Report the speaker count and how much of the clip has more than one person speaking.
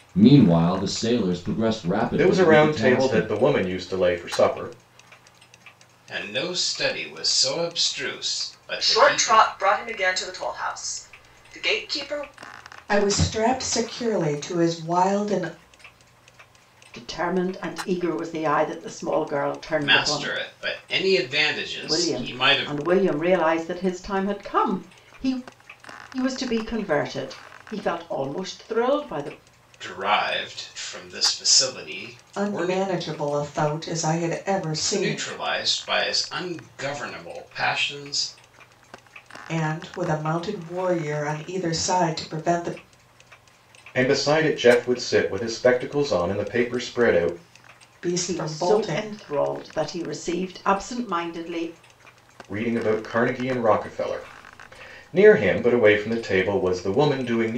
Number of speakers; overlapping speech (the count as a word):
six, about 9%